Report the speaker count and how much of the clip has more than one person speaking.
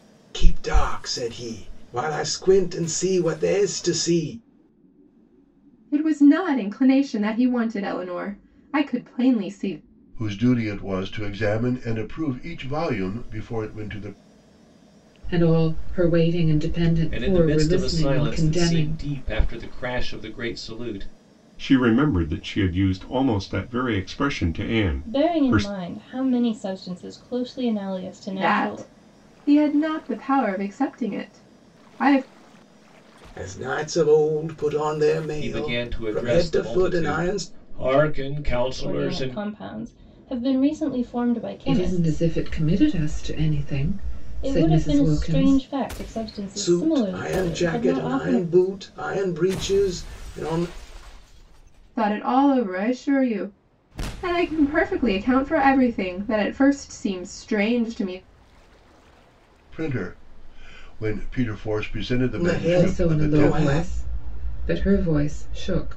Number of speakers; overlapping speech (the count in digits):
7, about 17%